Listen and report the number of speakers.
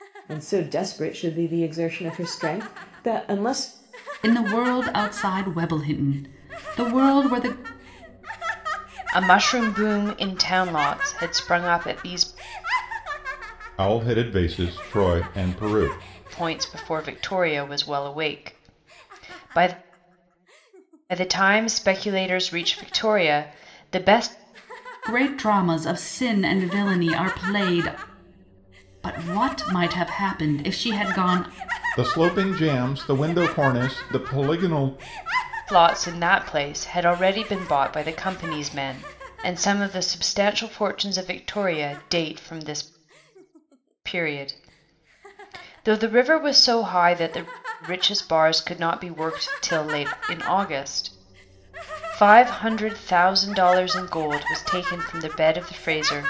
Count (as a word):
four